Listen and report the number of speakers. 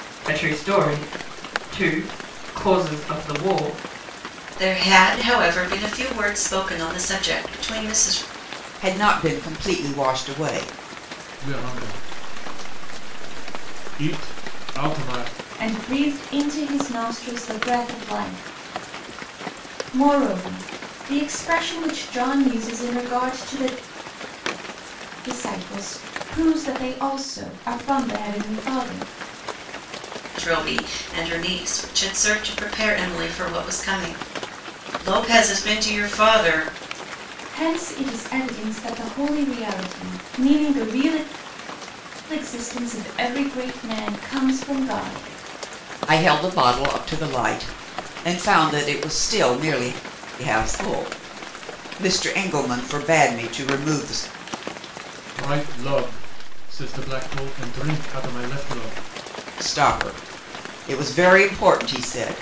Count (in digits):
5